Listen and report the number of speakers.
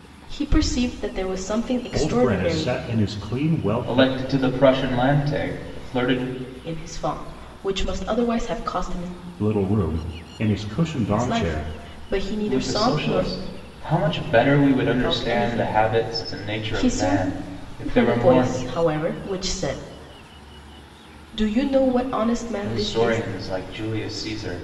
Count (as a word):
three